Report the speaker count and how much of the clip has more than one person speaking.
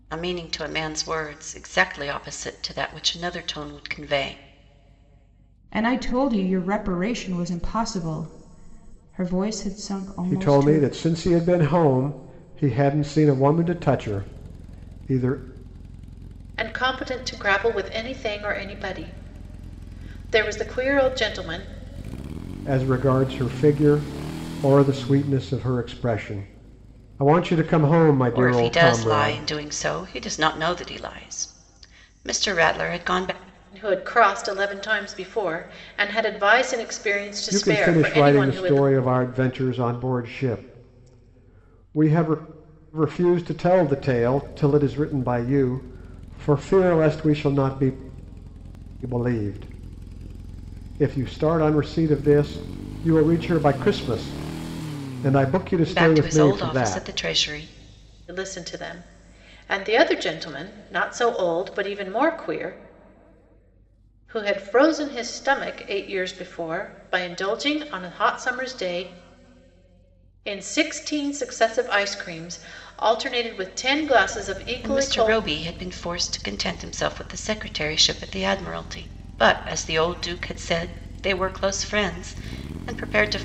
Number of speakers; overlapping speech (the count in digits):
4, about 6%